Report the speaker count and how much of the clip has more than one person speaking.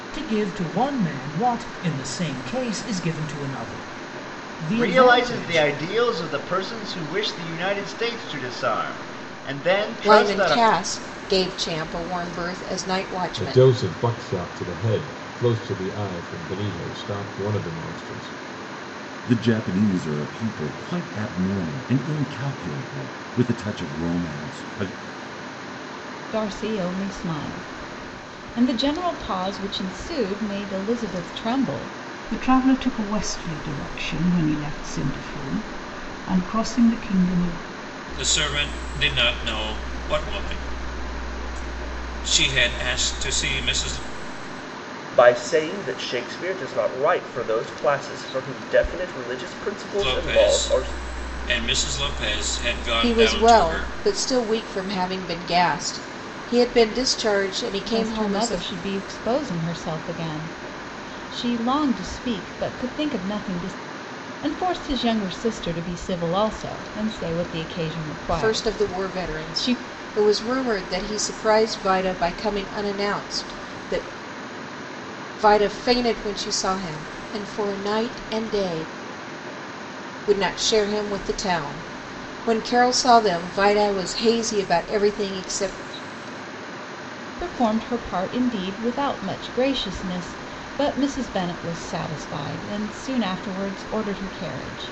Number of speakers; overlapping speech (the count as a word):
nine, about 7%